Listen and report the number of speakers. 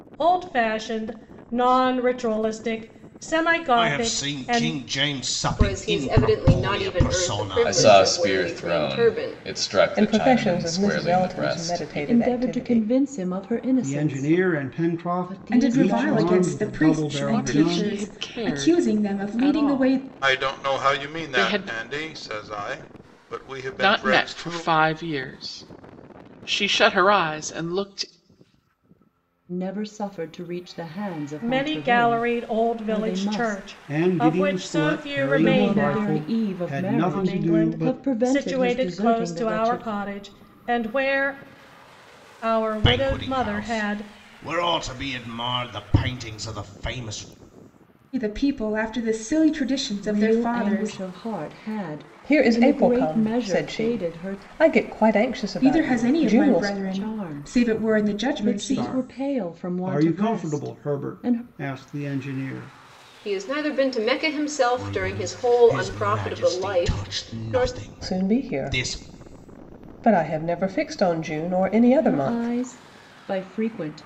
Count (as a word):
ten